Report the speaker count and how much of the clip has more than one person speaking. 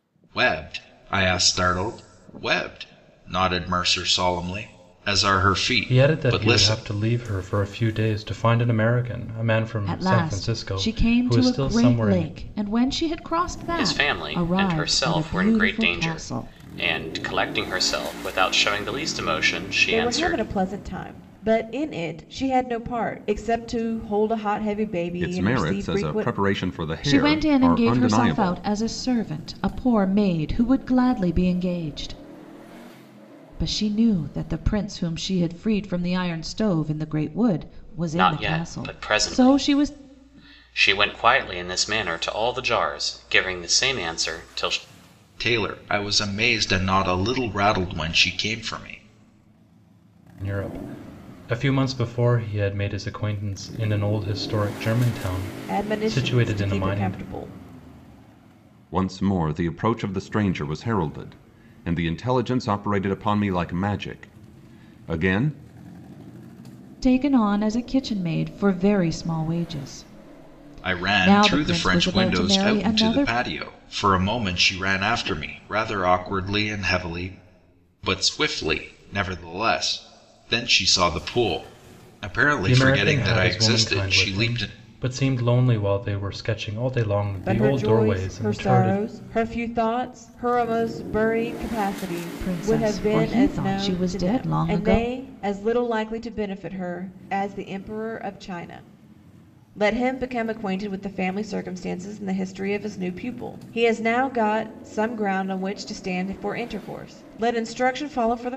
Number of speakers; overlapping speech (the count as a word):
six, about 21%